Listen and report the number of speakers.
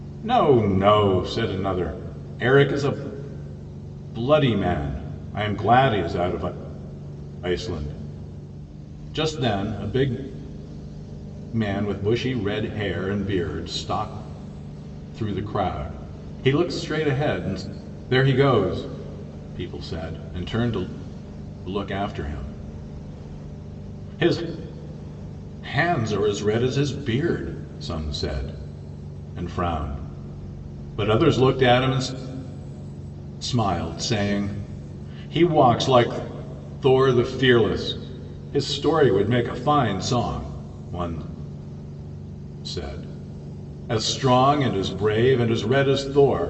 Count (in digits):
1